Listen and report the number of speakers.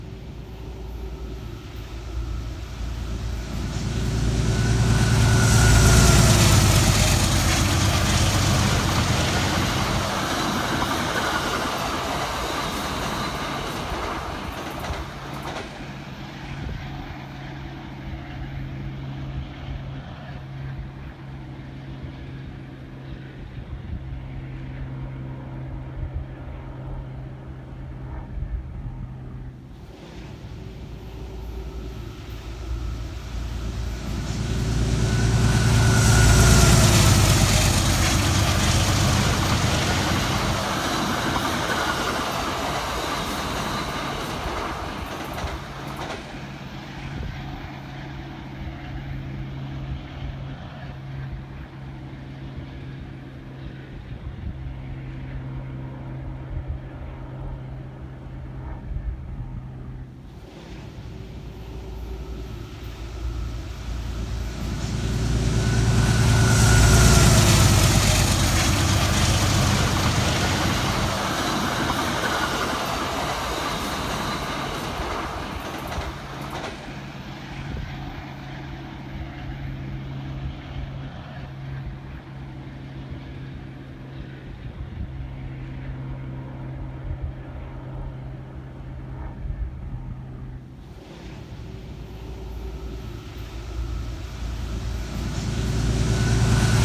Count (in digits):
0